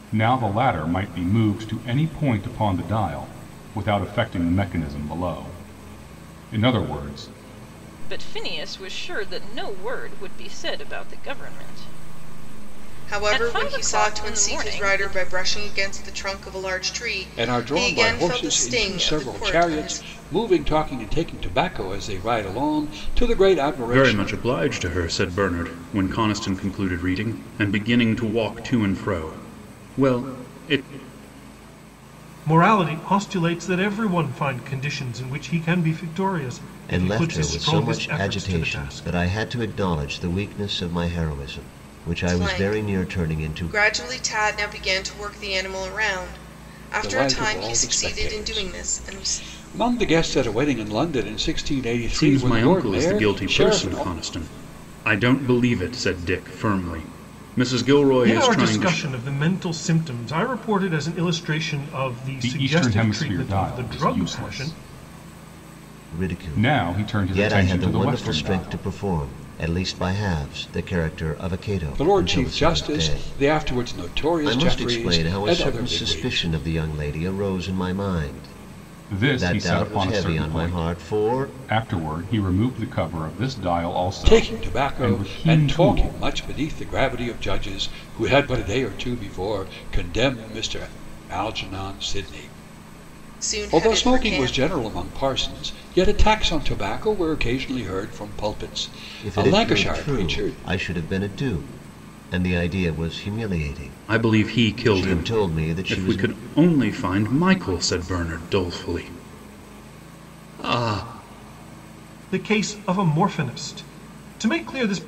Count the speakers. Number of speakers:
seven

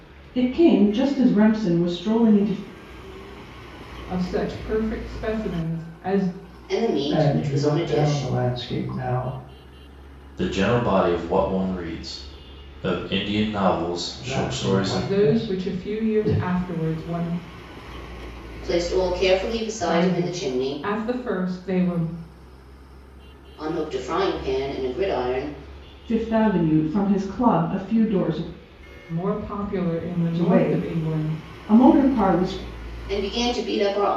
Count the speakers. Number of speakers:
five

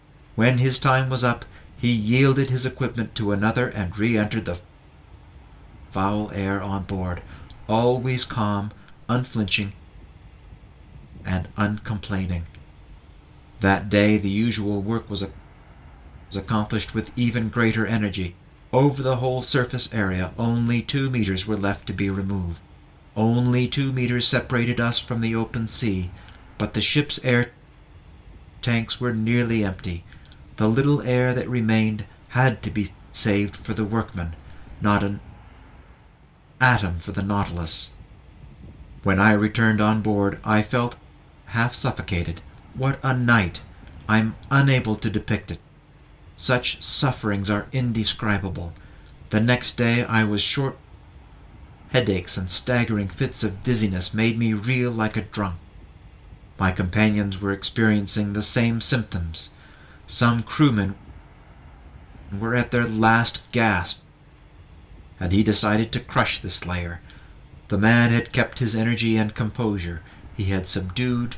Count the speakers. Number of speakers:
one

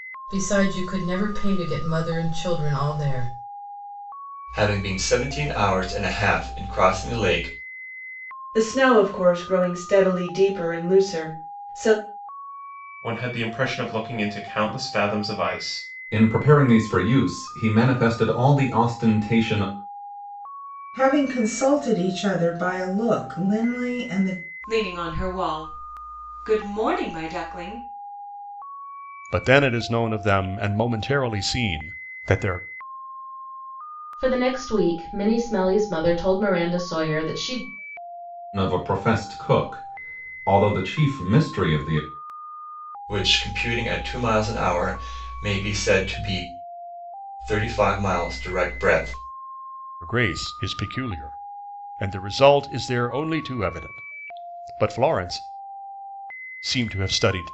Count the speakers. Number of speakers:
nine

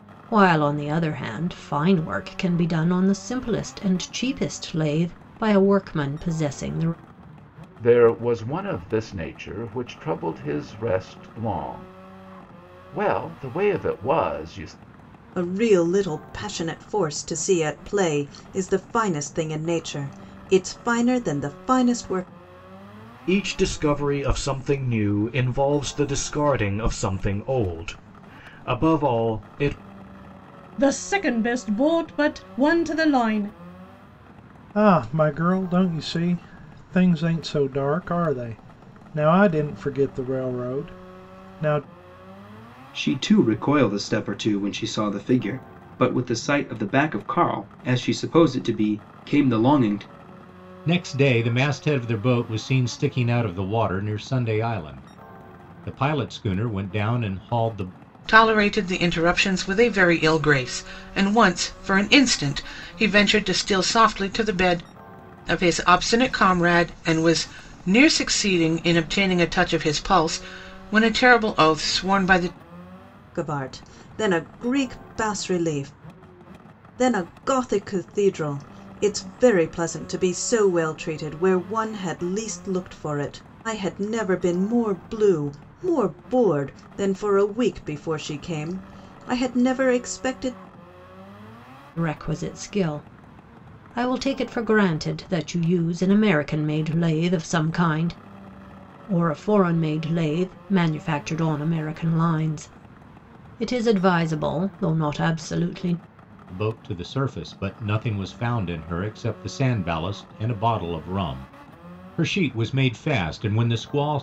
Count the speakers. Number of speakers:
nine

